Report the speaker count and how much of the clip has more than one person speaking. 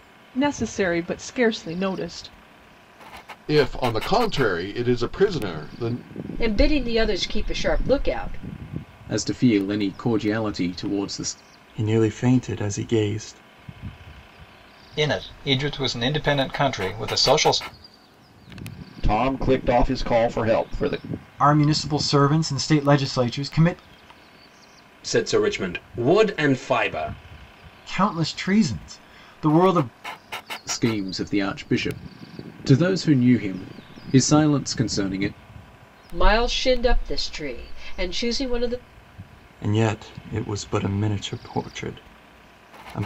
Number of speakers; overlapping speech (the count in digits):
9, no overlap